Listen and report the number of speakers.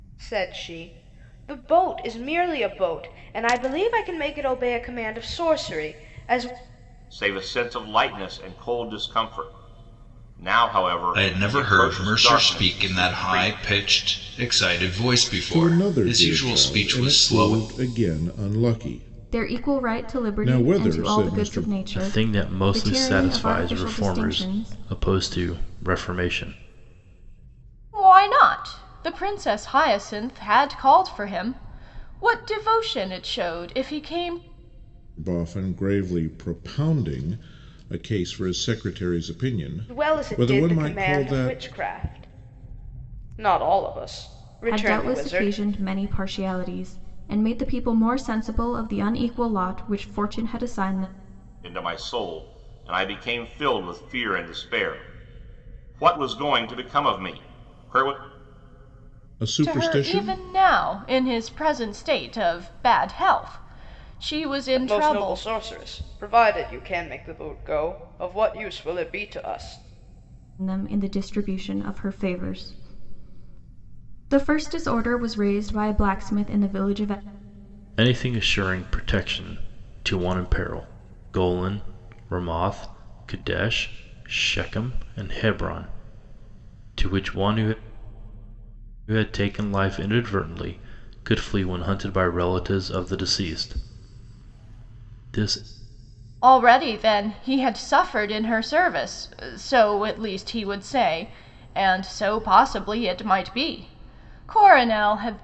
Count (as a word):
seven